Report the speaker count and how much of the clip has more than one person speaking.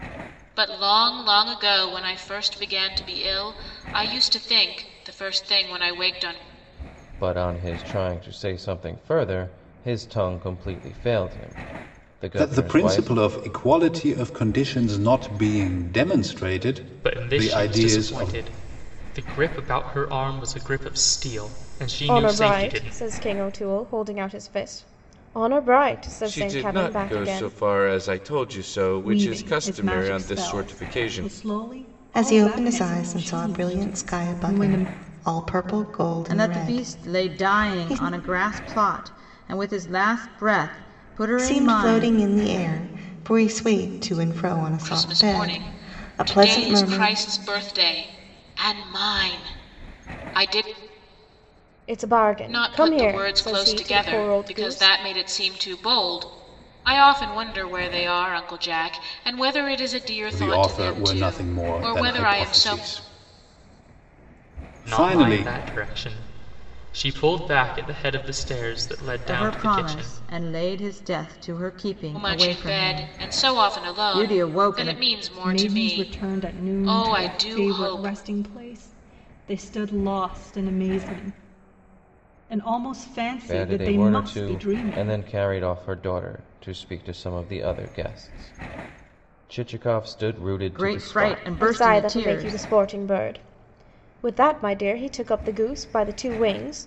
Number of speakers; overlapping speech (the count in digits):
9, about 31%